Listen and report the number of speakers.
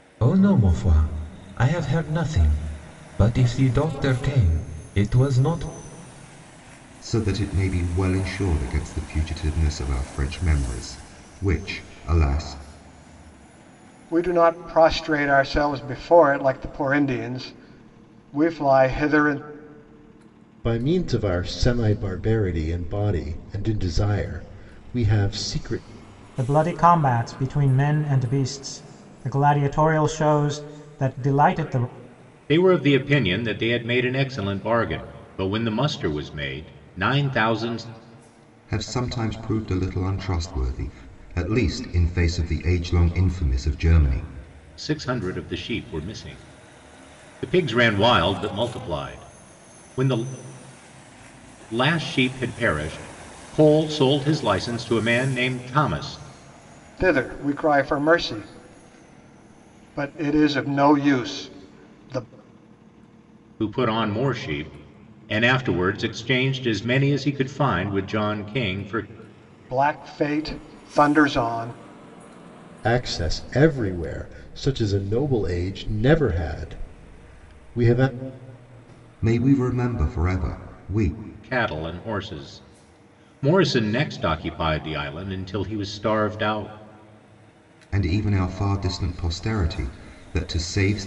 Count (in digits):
6